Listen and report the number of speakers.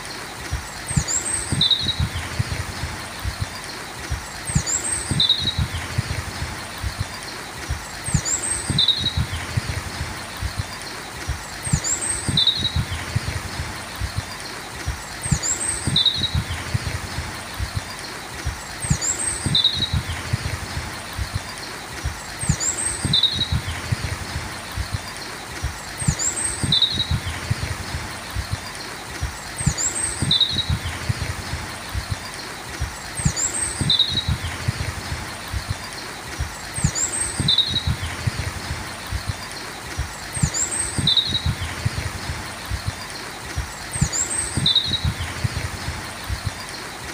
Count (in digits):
0